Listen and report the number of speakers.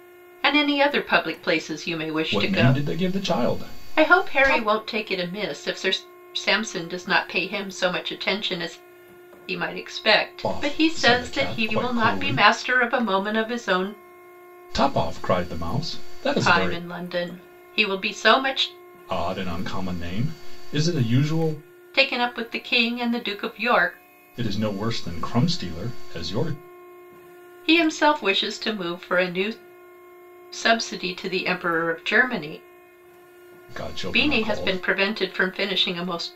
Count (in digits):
2